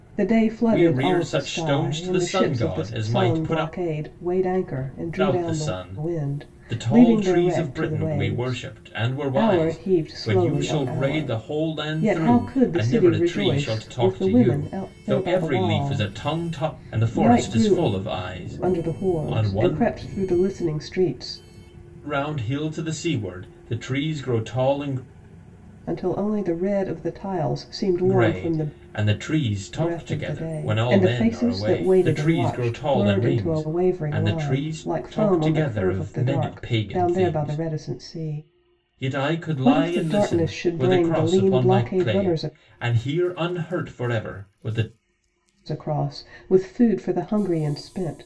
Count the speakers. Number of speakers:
two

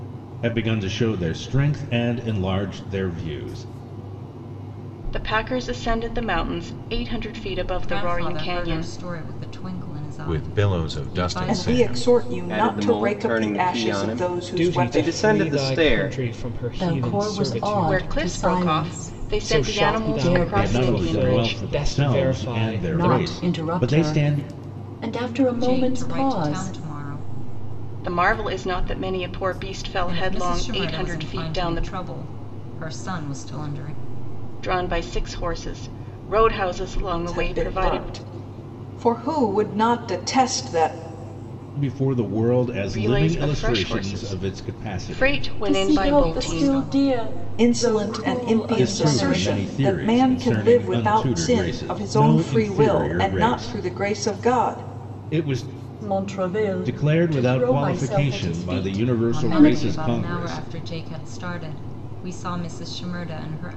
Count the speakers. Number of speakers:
eight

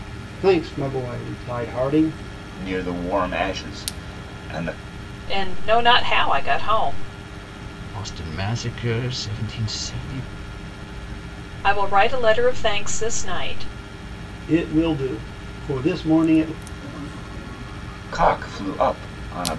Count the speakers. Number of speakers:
four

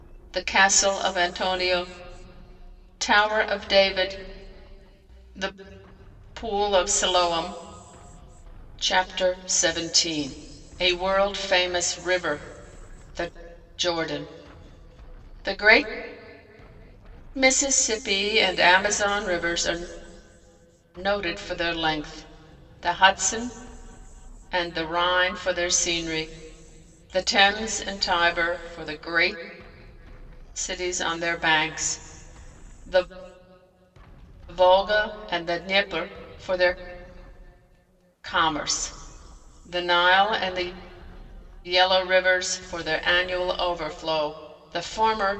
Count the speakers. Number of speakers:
one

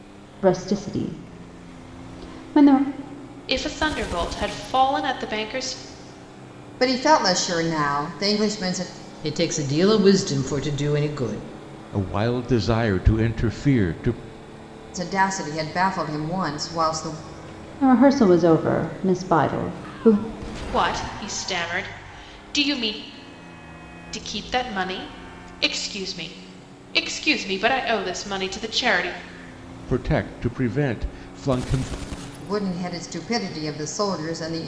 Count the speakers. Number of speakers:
five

